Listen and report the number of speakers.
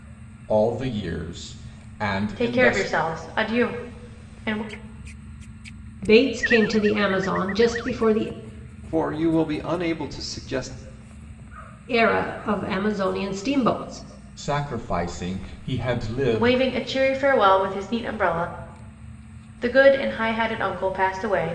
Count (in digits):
4